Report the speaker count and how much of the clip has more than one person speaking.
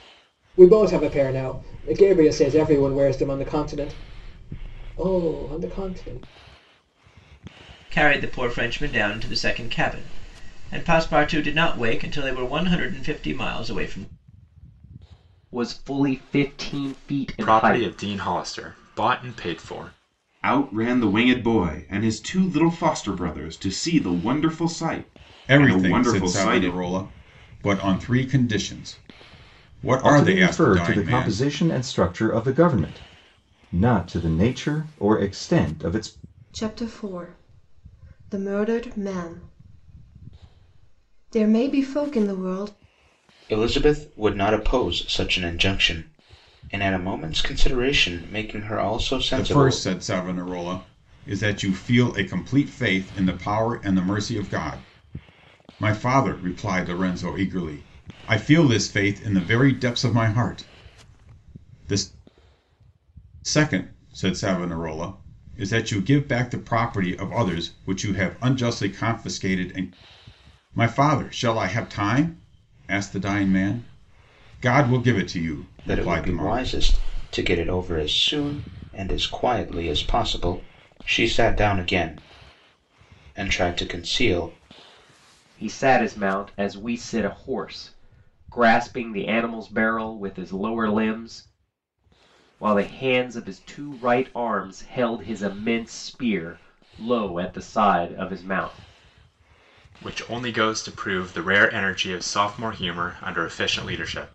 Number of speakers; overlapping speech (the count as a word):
nine, about 5%